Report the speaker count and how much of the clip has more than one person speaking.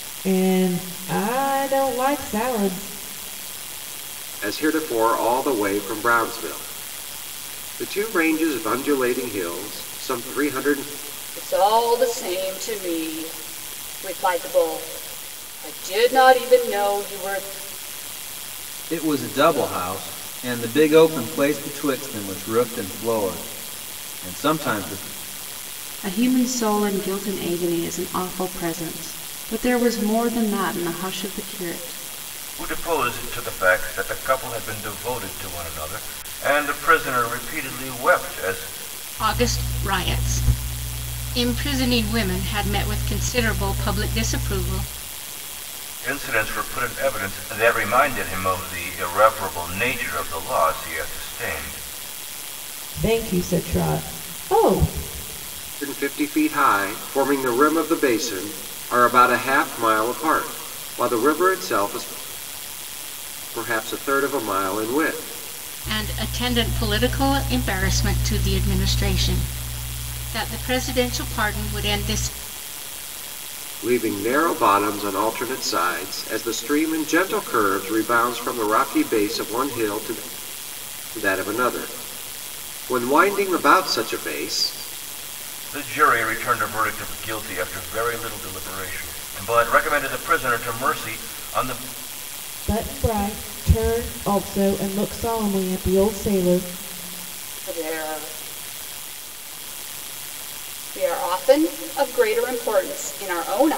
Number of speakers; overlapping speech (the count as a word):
seven, no overlap